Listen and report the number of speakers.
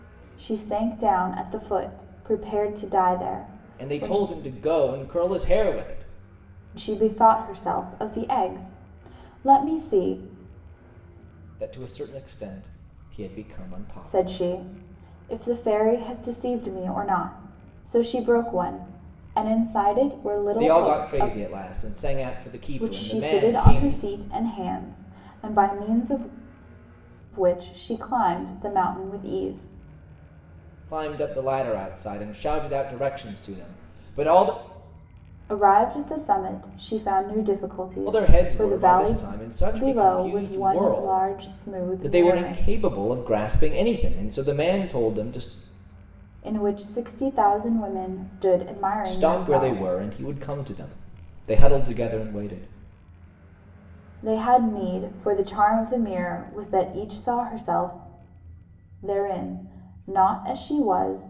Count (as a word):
two